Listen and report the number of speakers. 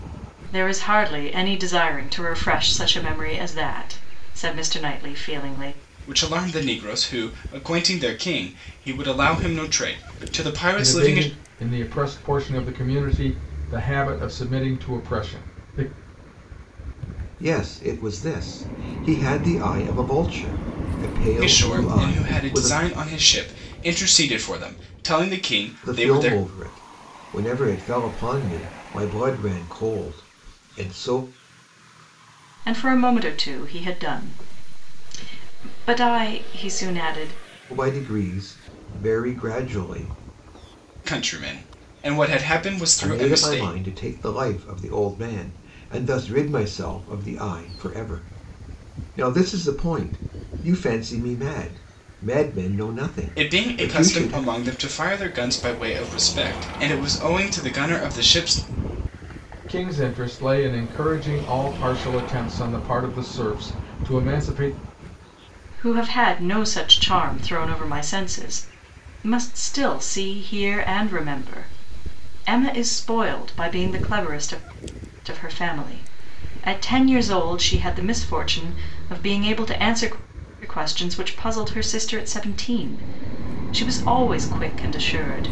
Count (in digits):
4